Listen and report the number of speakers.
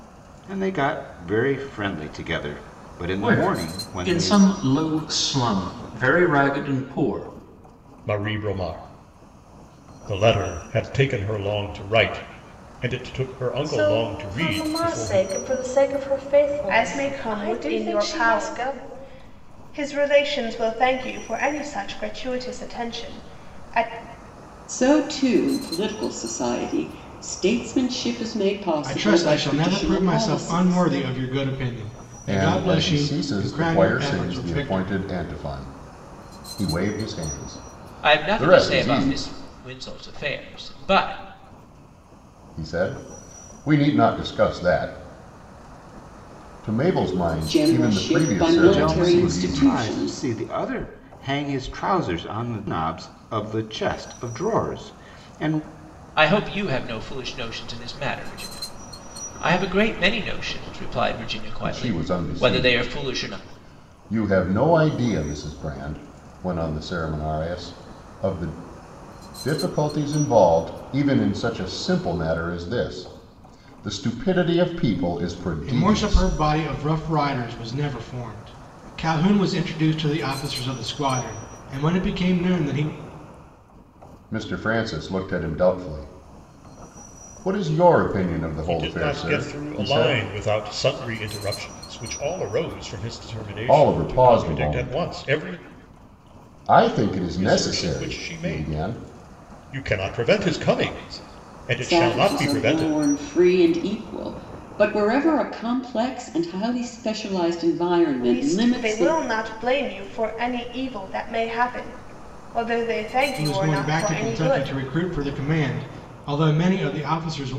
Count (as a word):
nine